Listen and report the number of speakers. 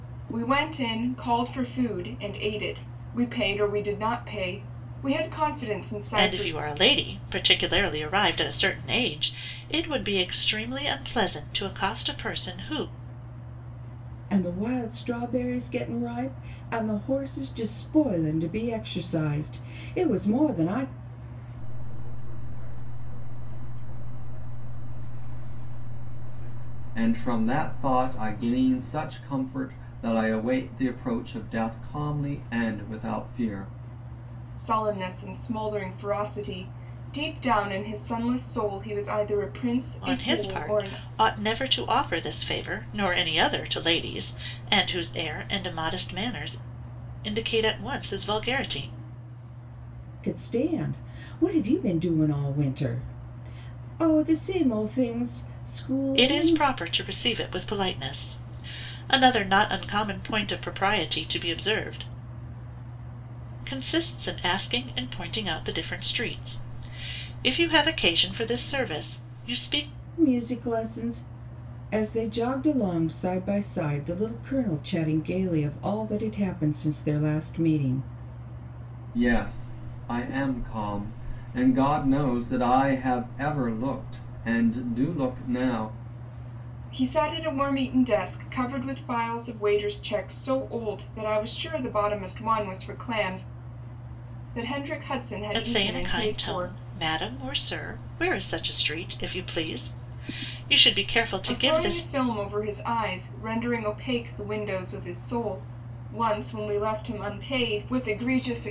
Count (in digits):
5